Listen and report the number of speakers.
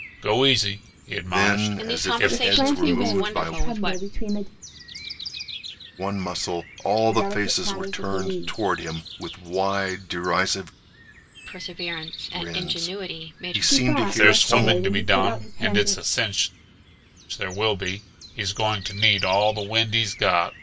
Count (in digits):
4